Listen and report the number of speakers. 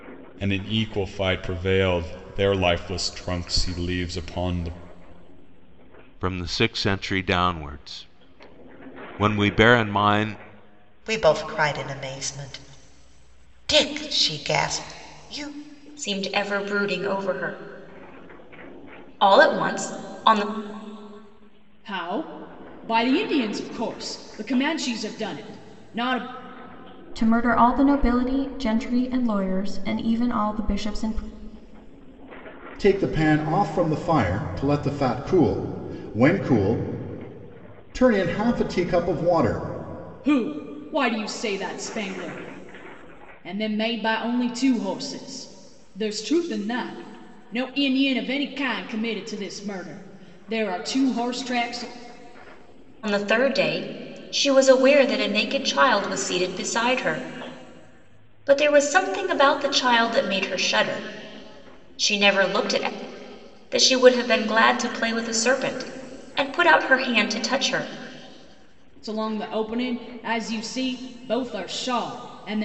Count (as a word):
seven